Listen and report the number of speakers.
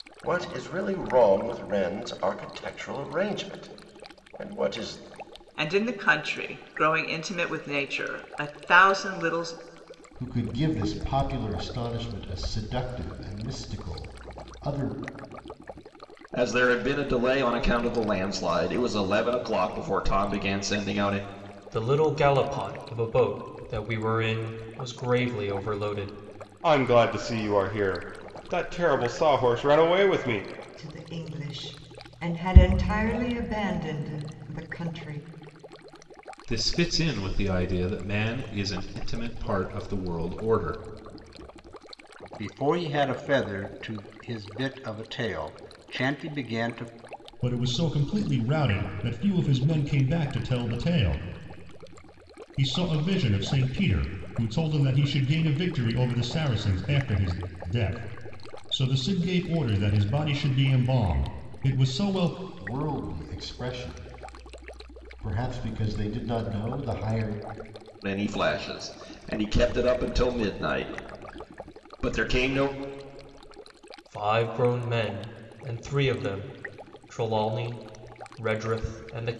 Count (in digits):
10